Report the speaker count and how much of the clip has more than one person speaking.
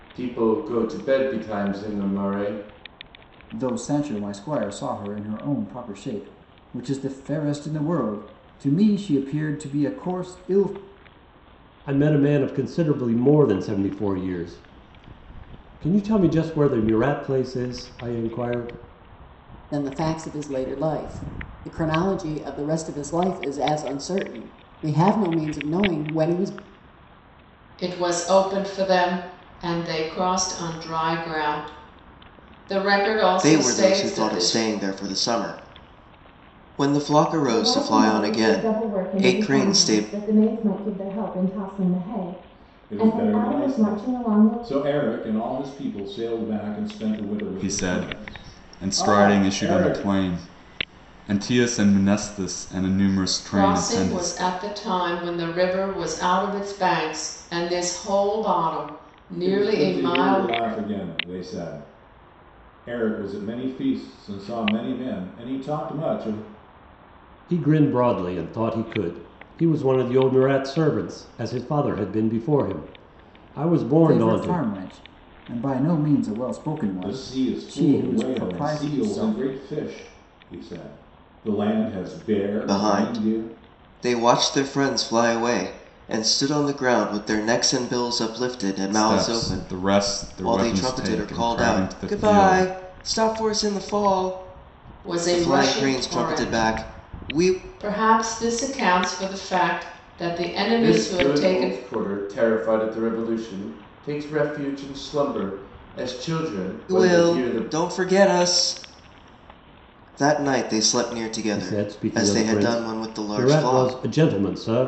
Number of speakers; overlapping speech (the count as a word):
nine, about 21%